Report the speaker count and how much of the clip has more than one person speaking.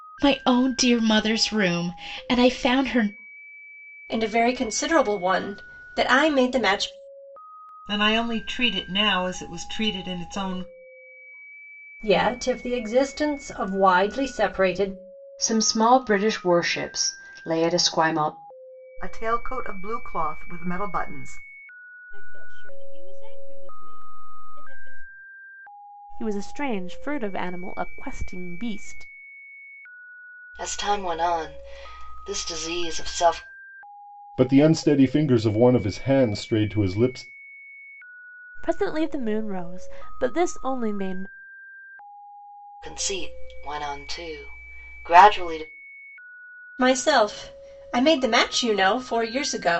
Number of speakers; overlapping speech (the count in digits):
10, no overlap